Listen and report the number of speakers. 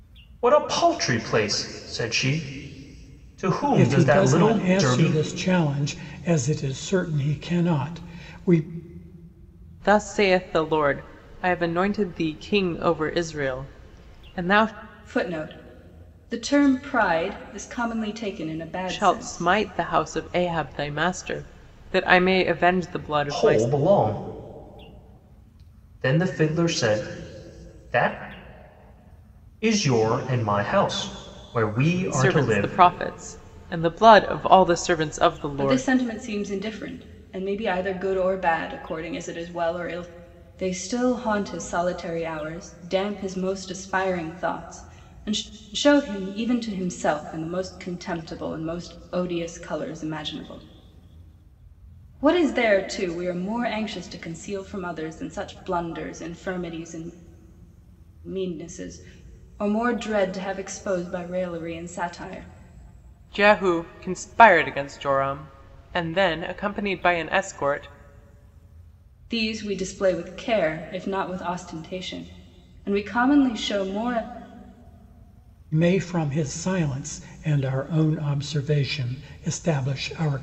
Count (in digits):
4